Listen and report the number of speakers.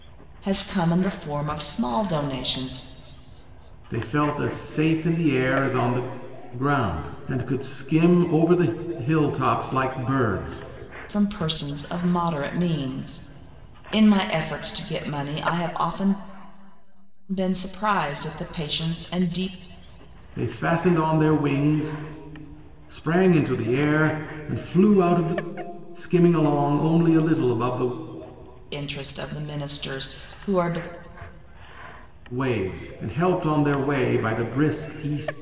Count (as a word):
two